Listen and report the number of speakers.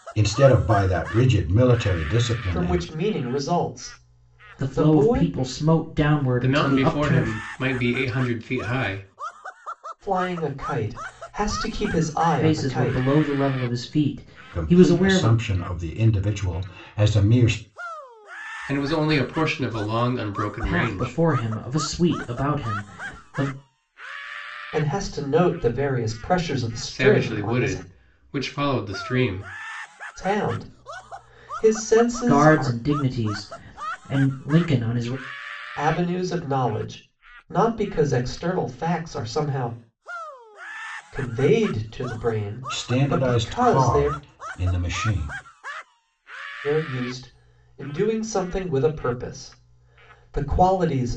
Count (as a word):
four